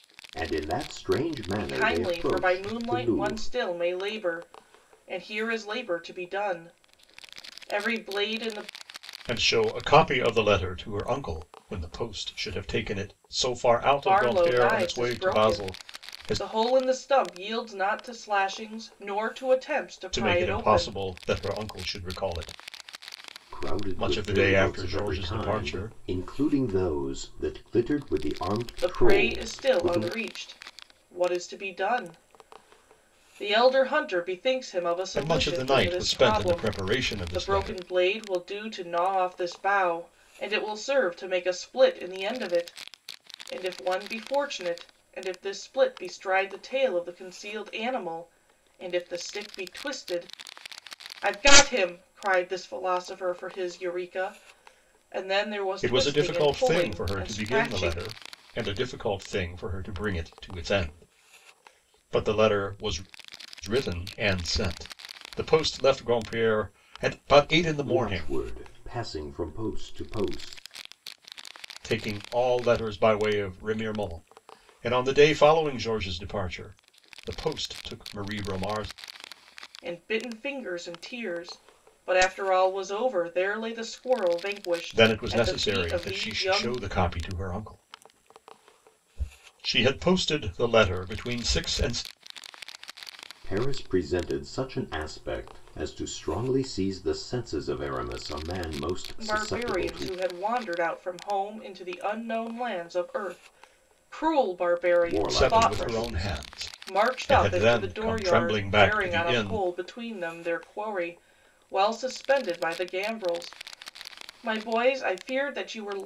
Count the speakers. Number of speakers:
3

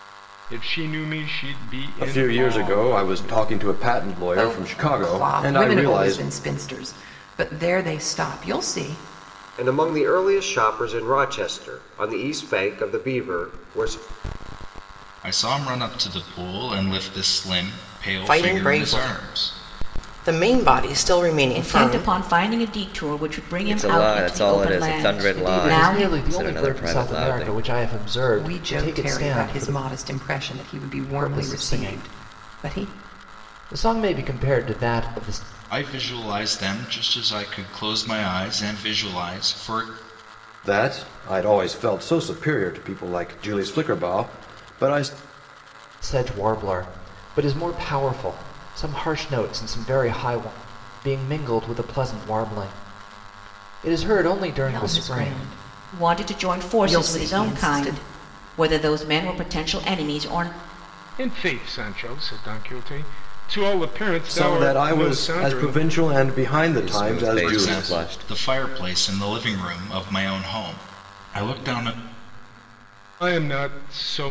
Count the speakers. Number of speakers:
9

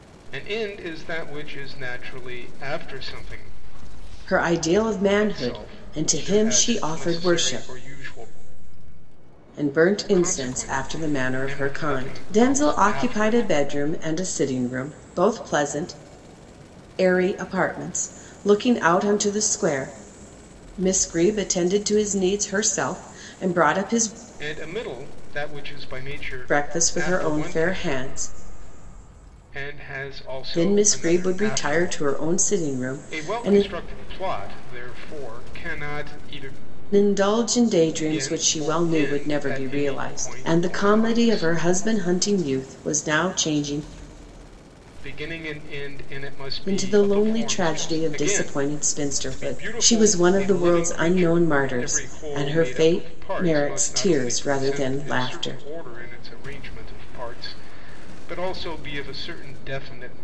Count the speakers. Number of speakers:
2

